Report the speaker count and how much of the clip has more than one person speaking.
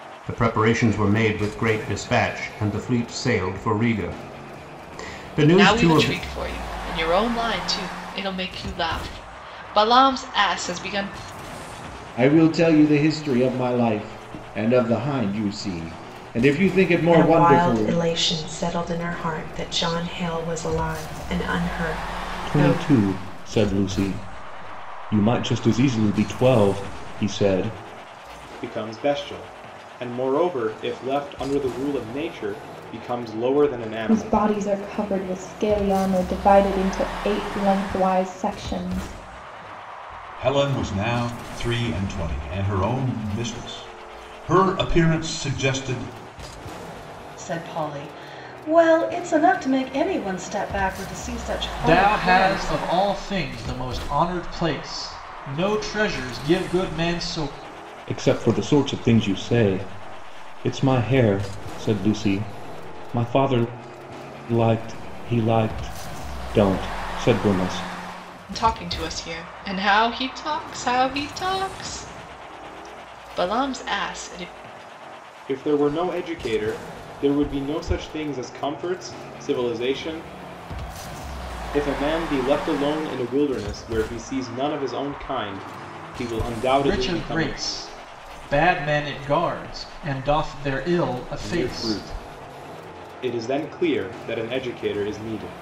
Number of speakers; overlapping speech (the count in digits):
10, about 5%